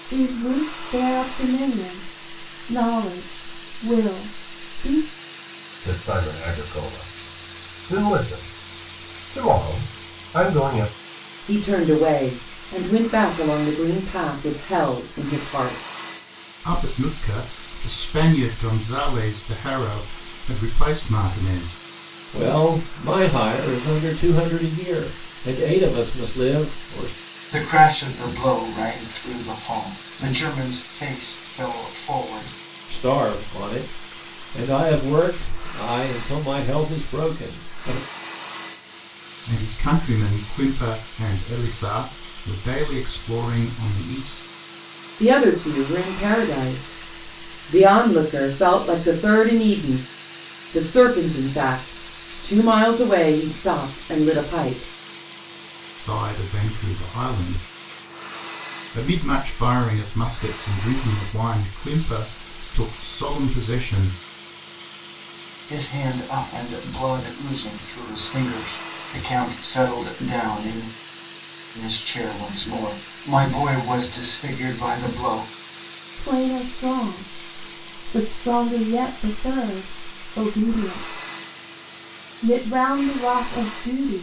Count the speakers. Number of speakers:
6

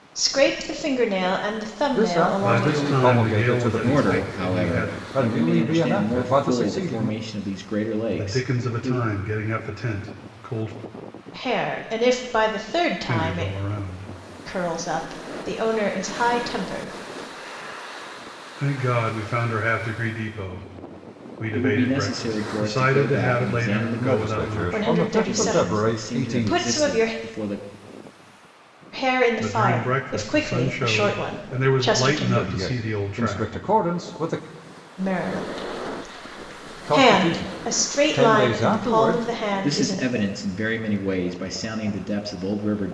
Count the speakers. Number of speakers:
4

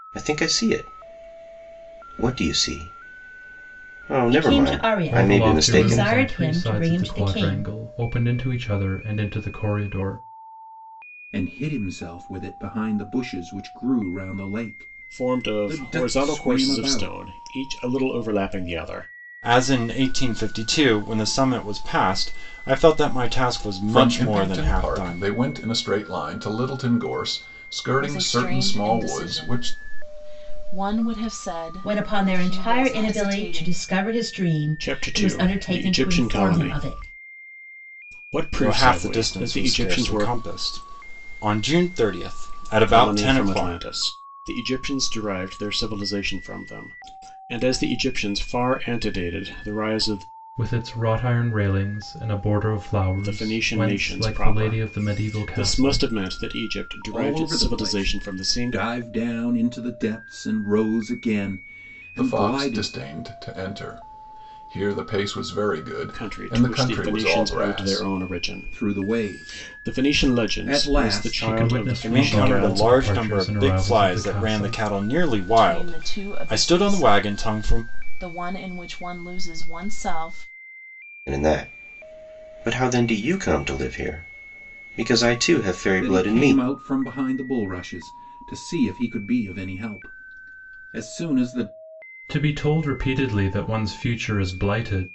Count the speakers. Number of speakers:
8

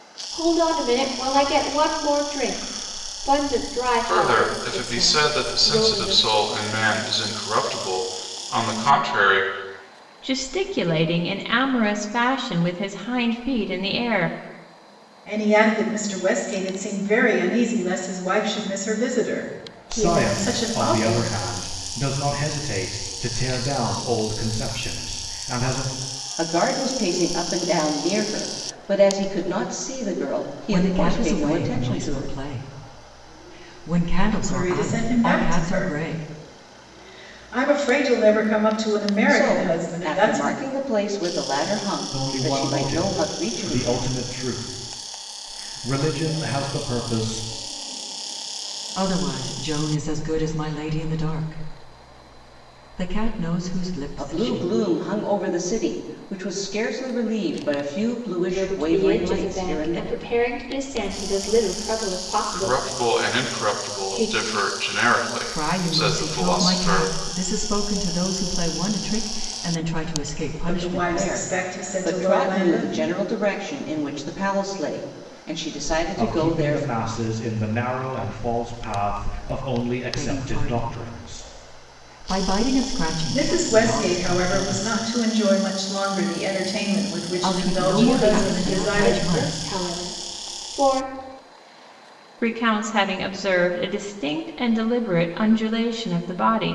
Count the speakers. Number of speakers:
7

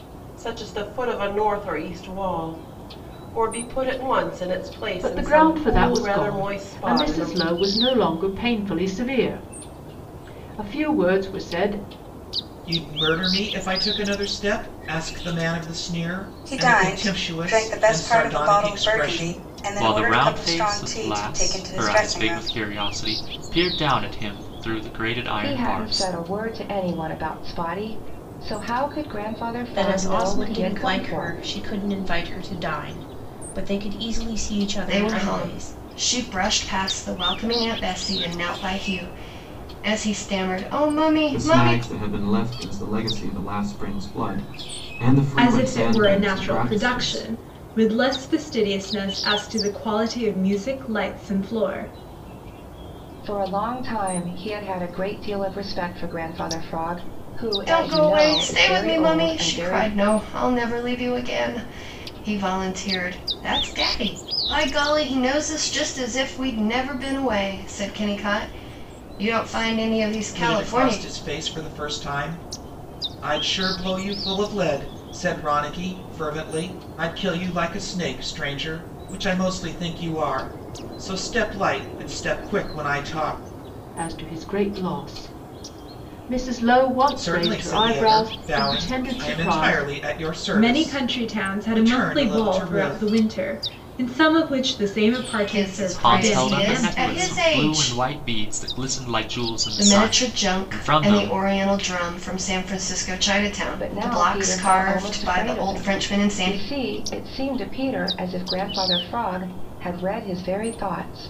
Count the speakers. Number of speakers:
10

